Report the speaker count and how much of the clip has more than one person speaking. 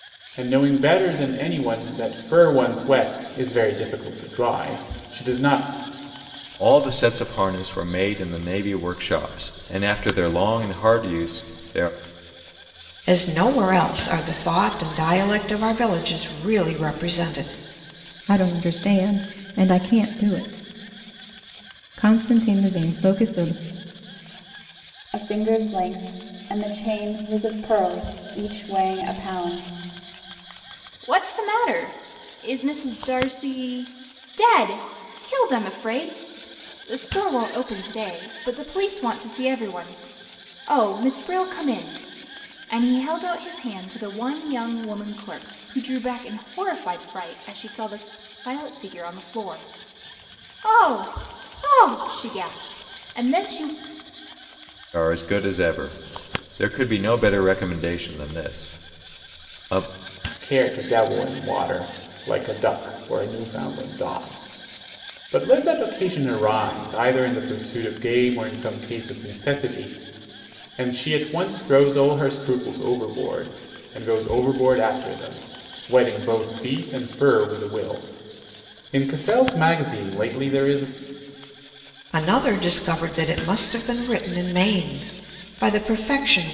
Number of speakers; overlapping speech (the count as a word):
six, no overlap